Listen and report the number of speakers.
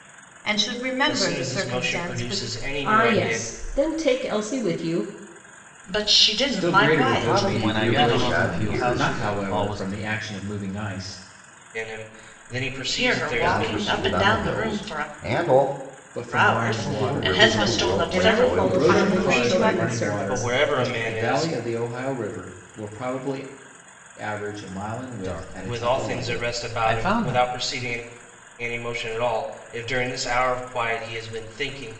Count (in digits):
7